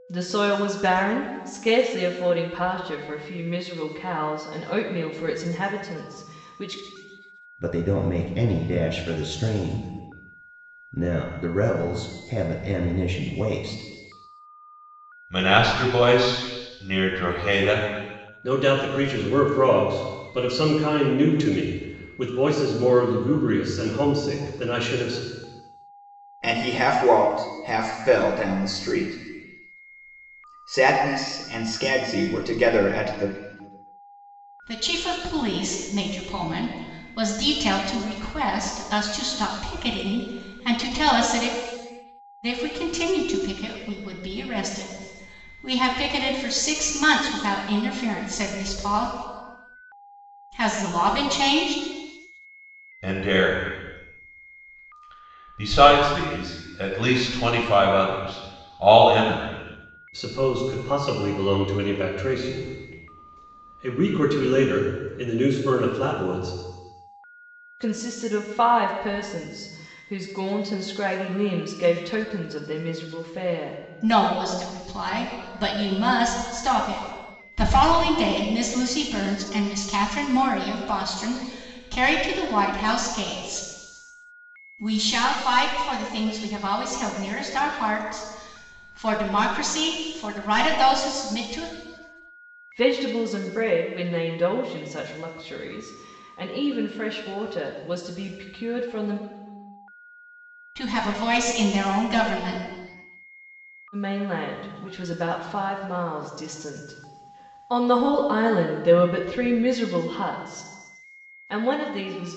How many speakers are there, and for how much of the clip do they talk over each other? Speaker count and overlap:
six, no overlap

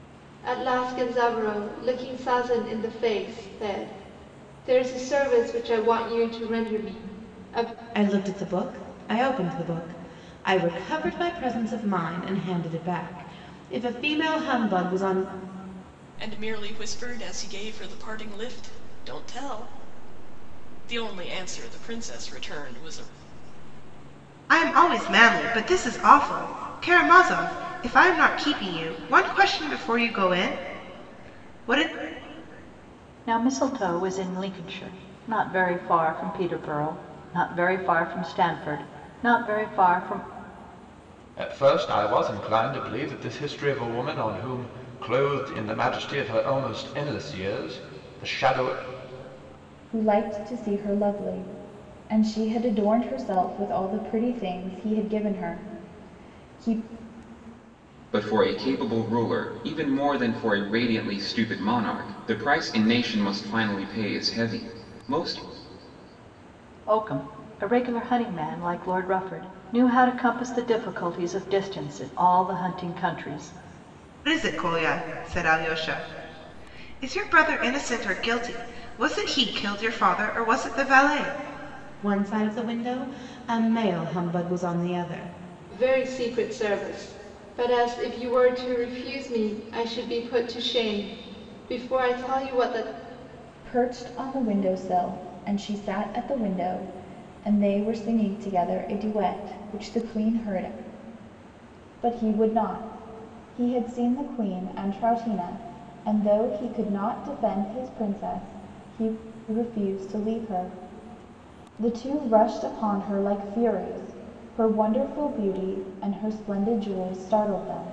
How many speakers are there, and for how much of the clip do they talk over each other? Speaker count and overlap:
eight, no overlap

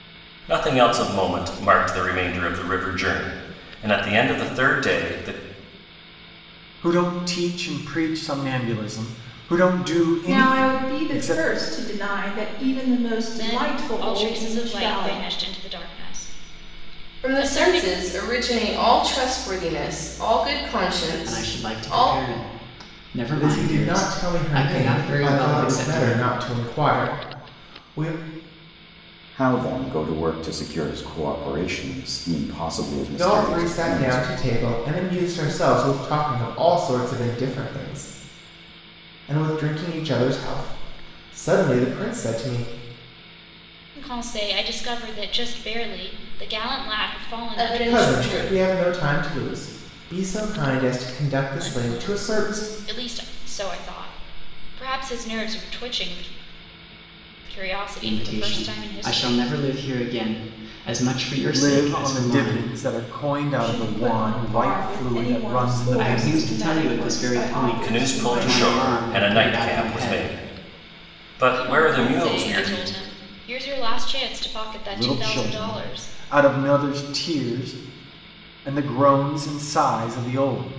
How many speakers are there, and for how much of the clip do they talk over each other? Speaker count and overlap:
eight, about 29%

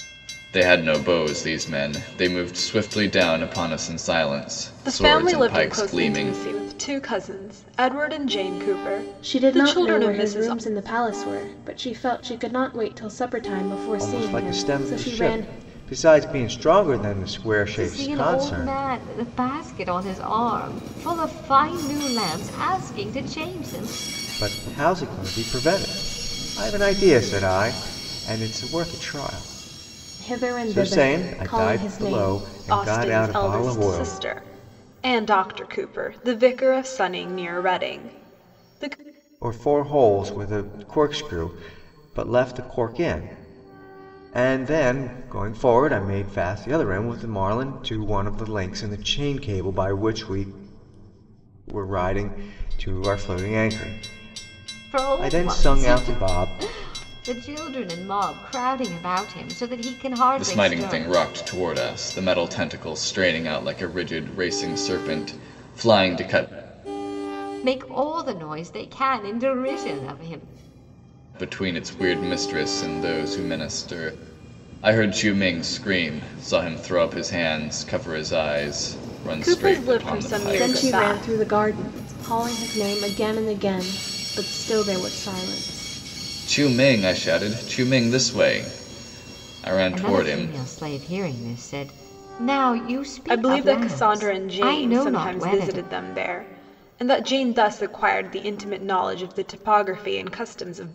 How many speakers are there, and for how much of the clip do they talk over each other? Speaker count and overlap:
five, about 17%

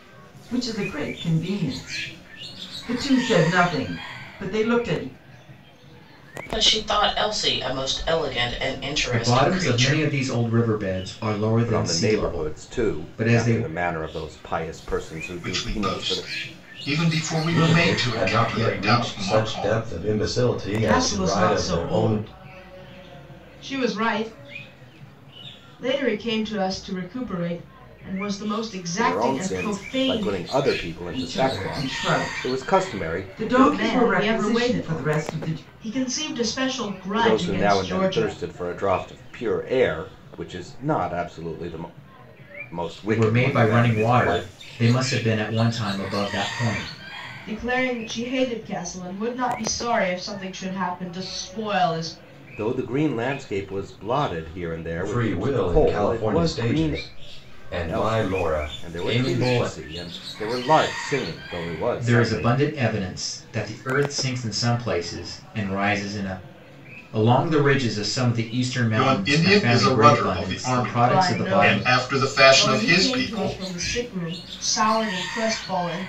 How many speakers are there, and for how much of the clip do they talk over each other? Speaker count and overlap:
seven, about 33%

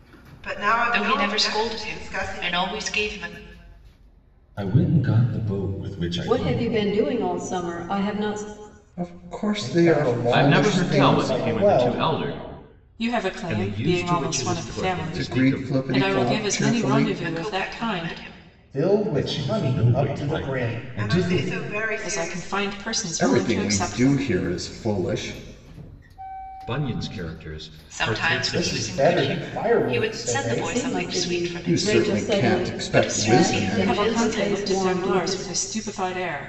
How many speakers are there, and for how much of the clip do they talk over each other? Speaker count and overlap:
nine, about 57%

